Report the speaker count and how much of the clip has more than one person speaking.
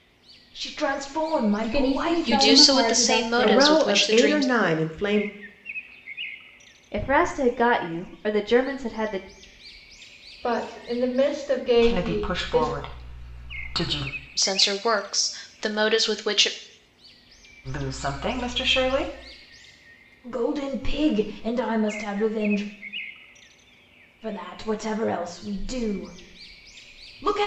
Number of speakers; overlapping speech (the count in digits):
7, about 14%